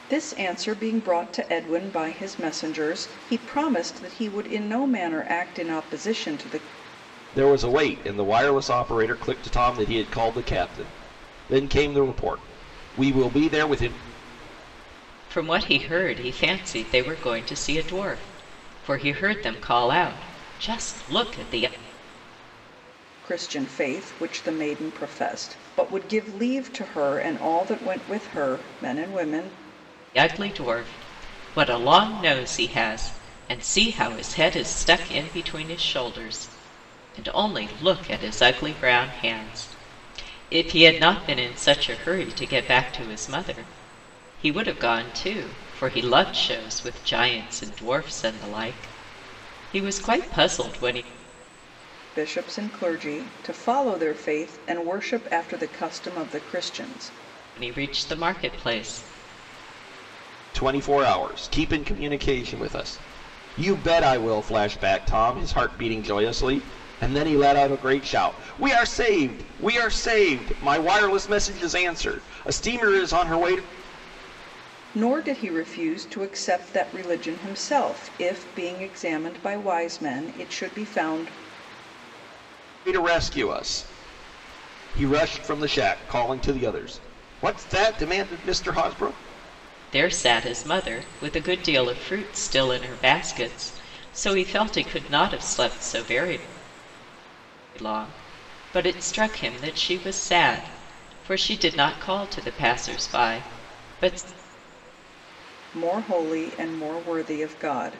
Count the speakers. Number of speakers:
three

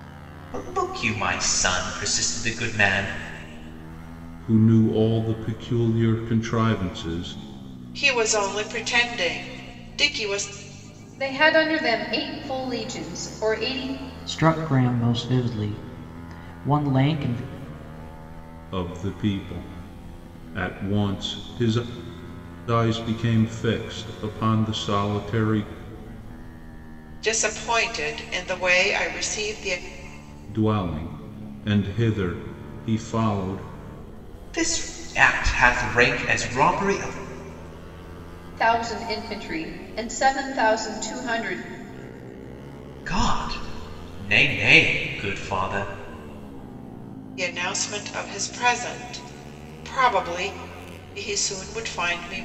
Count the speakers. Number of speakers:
five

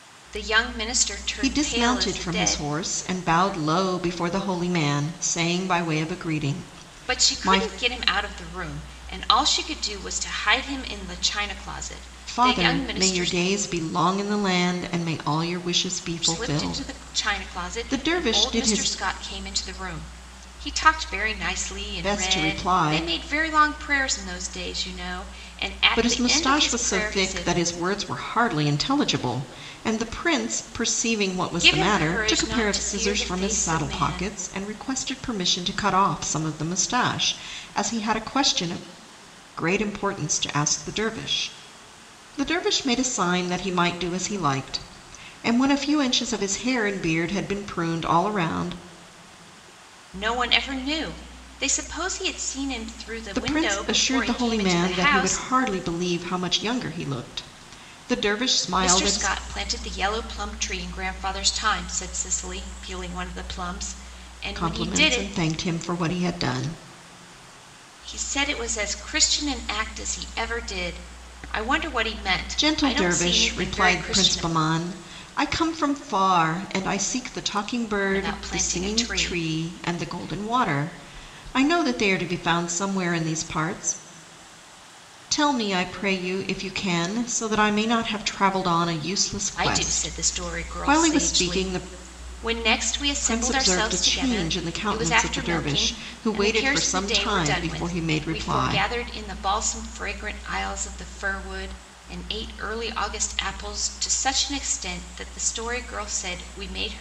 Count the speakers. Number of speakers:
two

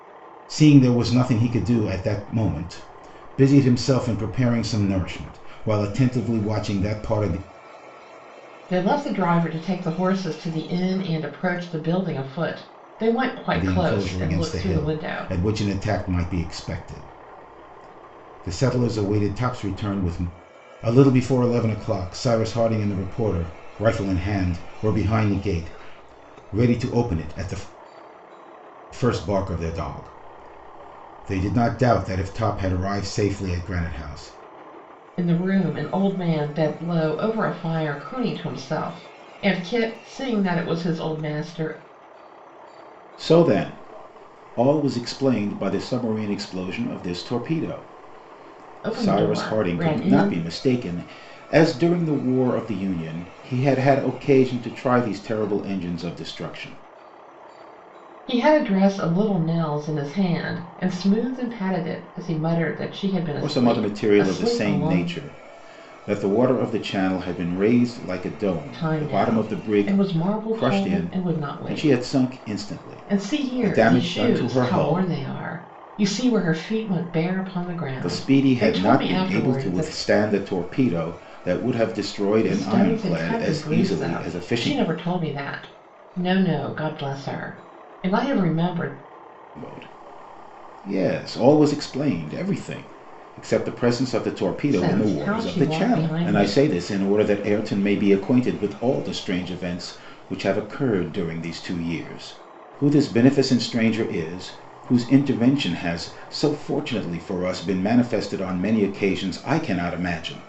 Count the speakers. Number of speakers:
two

